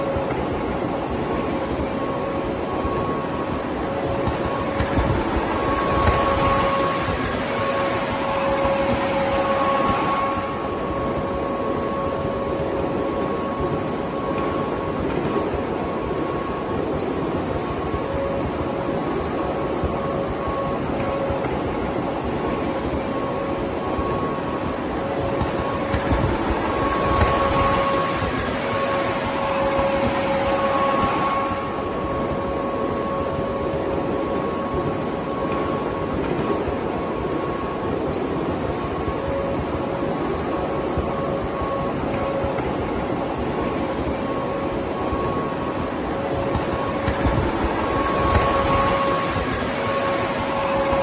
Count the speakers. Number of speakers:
0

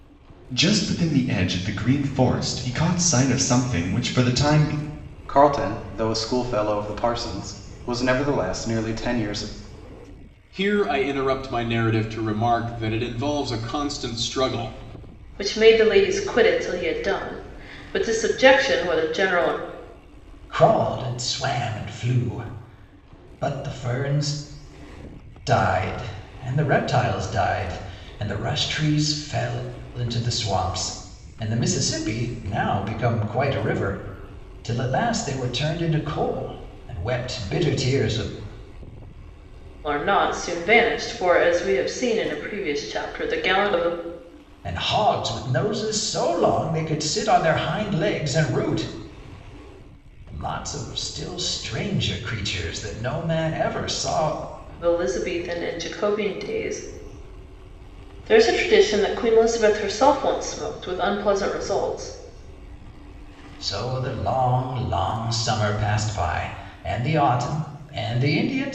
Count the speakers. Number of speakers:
5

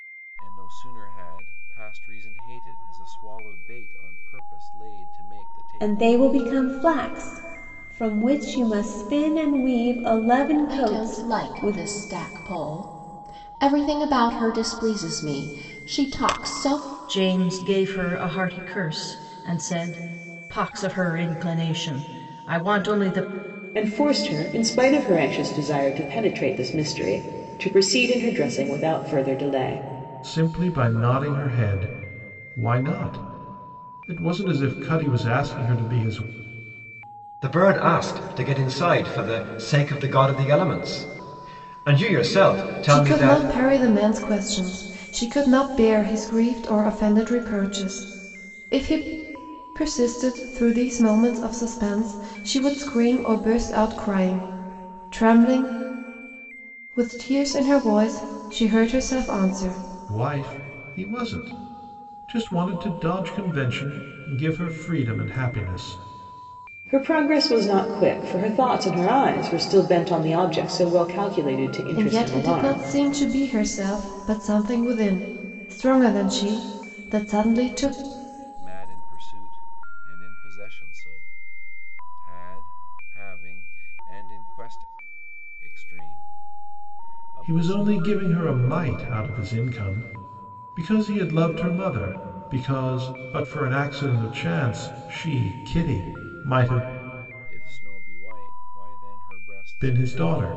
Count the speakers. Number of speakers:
8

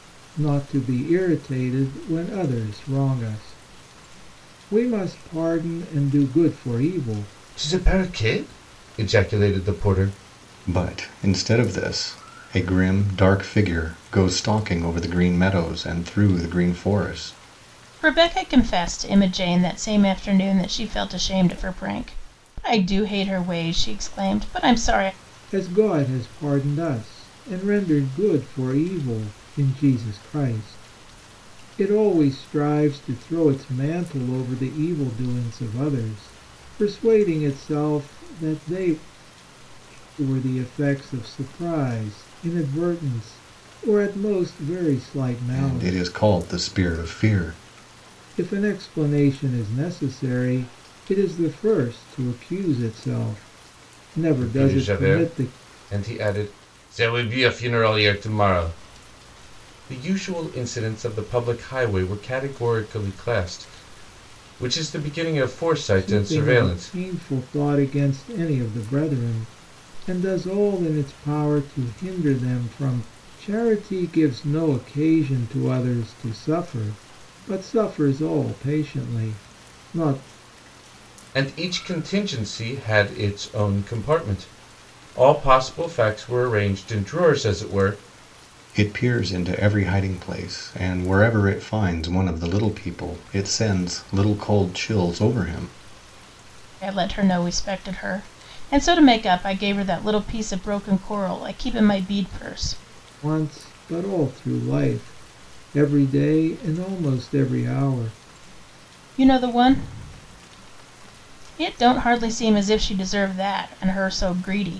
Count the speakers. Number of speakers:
4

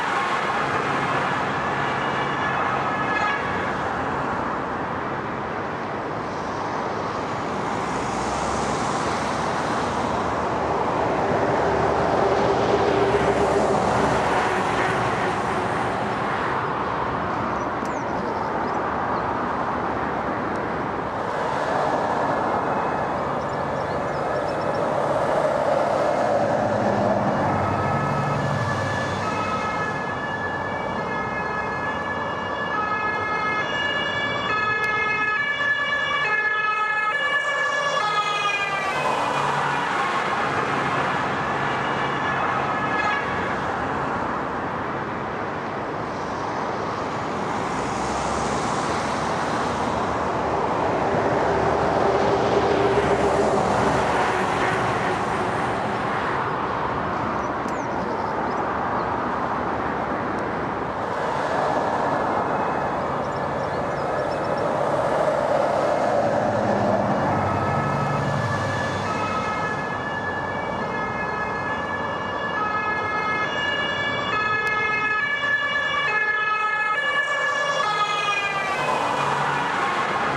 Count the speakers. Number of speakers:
0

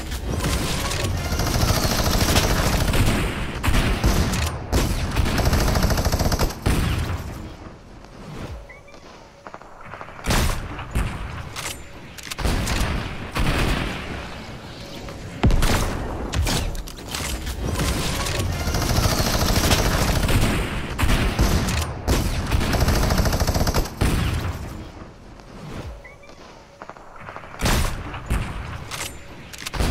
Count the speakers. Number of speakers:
0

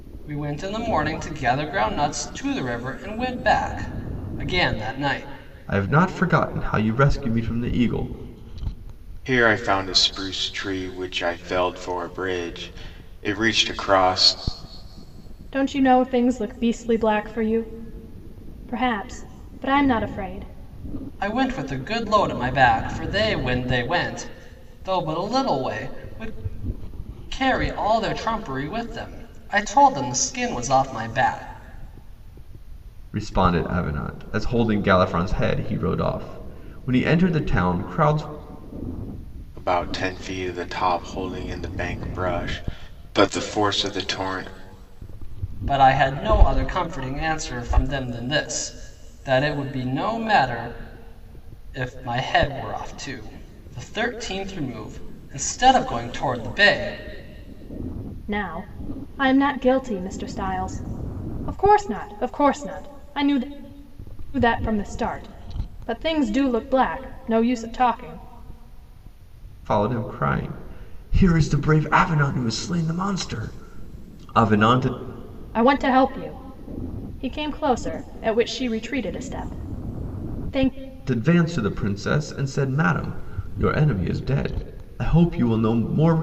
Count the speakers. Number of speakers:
4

